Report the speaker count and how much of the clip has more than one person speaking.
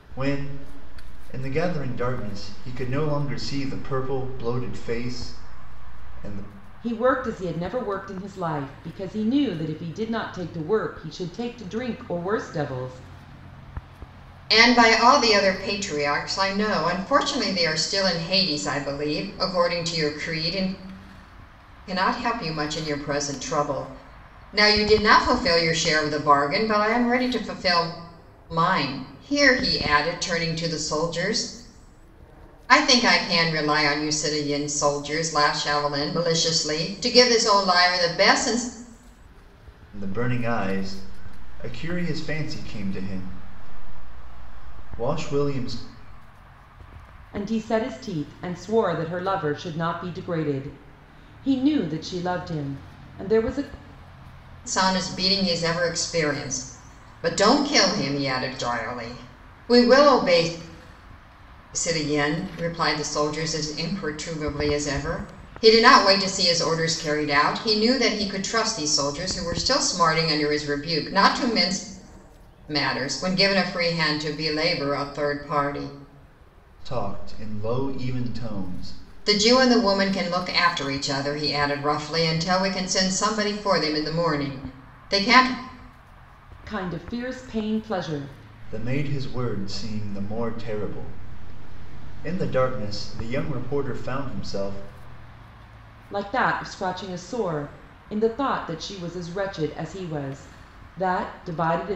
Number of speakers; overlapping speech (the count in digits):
3, no overlap